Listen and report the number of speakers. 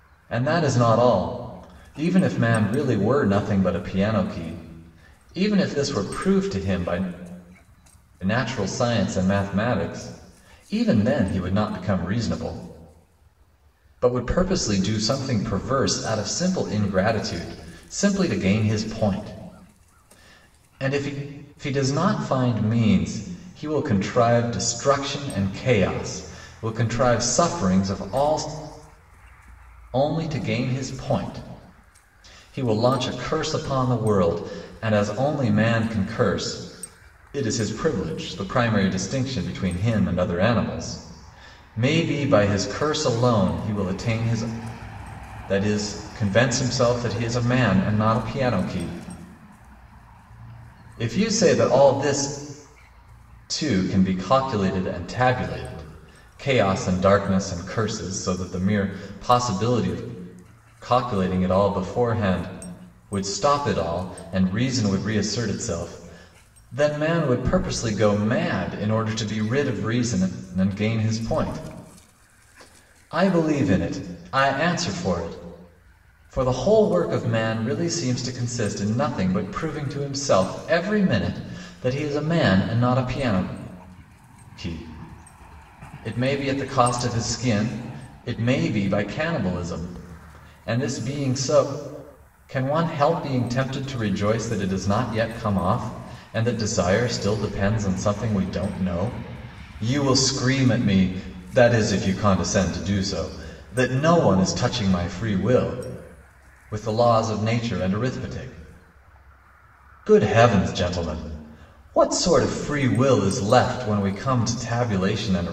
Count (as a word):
one